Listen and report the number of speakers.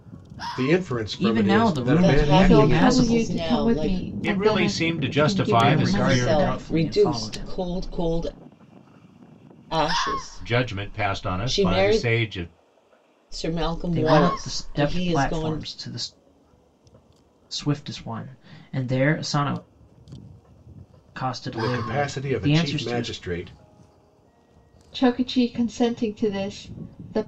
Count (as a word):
five